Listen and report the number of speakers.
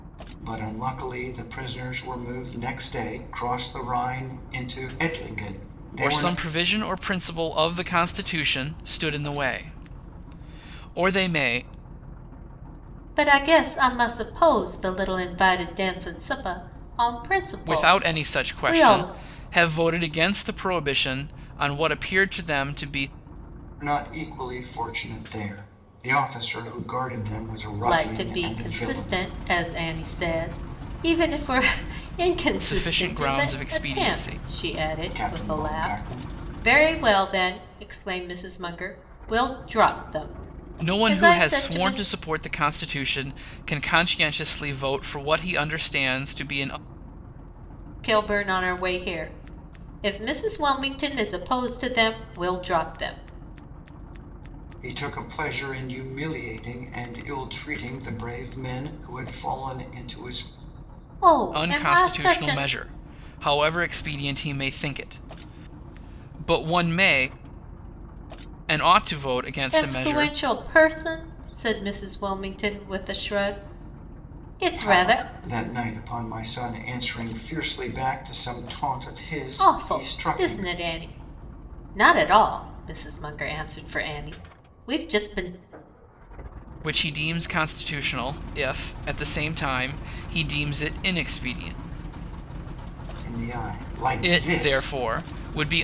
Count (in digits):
3